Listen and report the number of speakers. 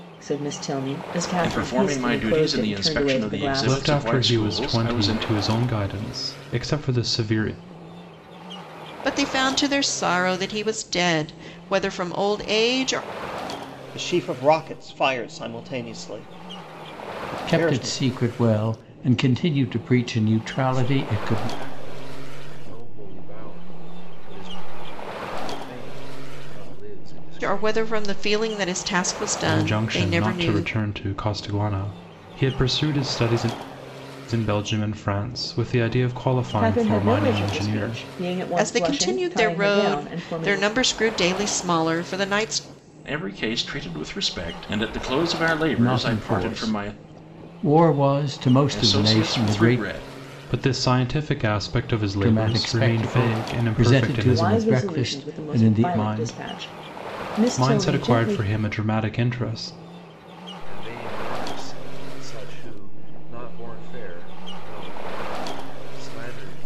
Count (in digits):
7